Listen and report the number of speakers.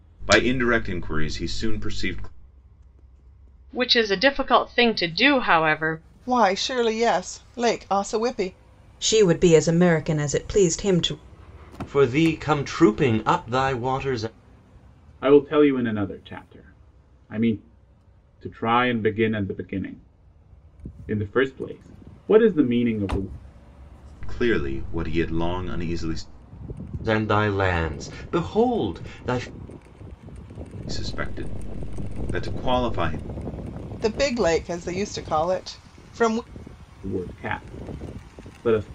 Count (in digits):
6